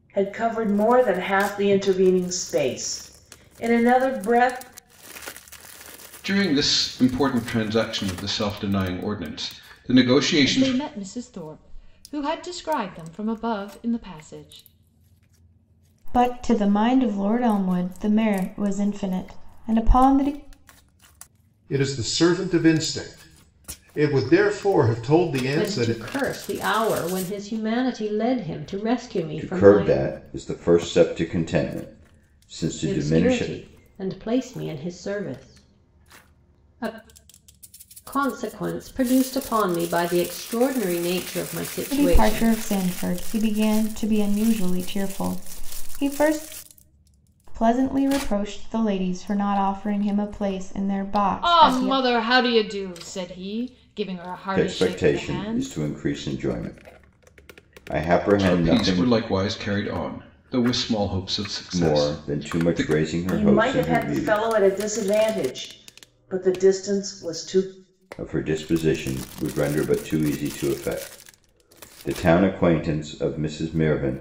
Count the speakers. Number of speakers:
seven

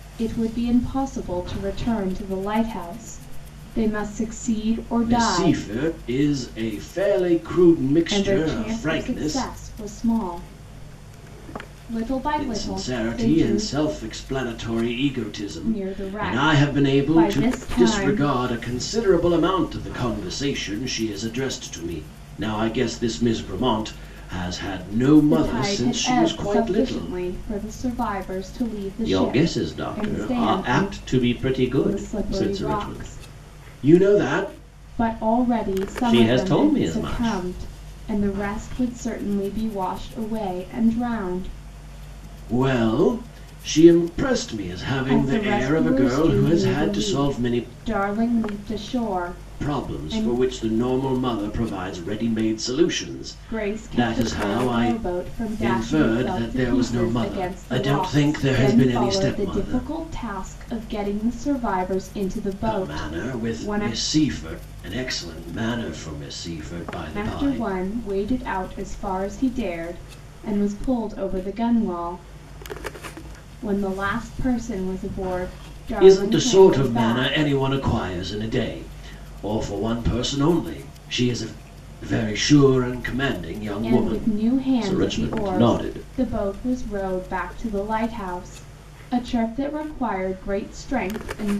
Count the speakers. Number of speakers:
two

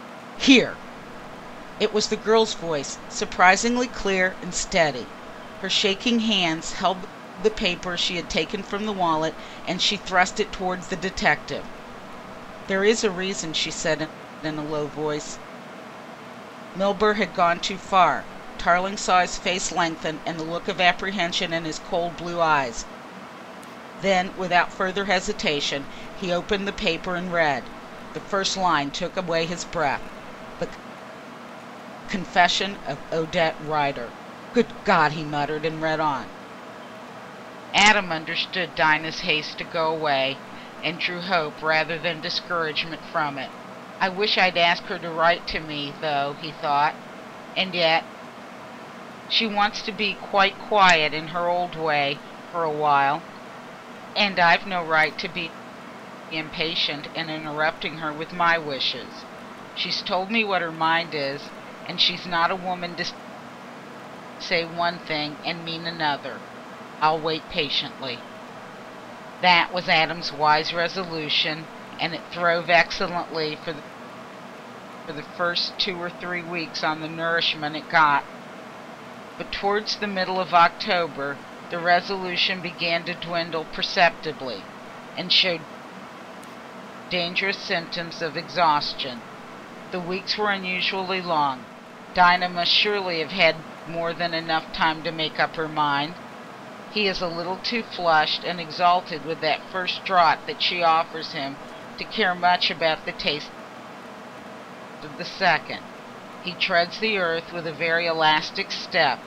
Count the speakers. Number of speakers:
one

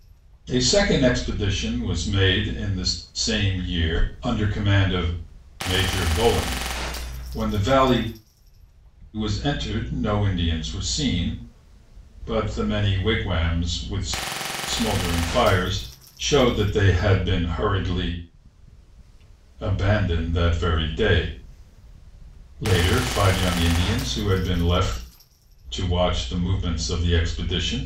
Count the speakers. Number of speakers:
one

